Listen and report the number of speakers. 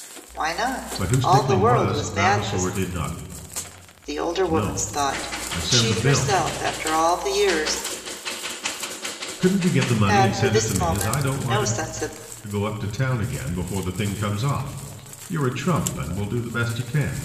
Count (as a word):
two